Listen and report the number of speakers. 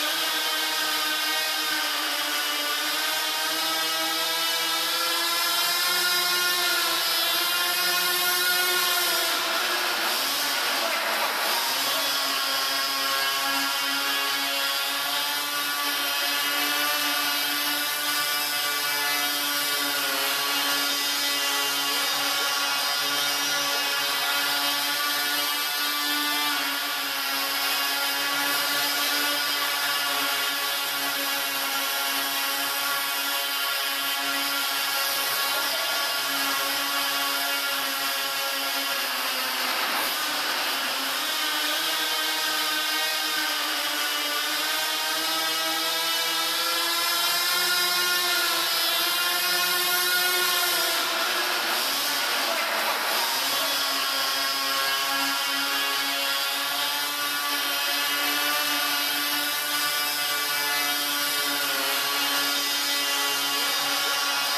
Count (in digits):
0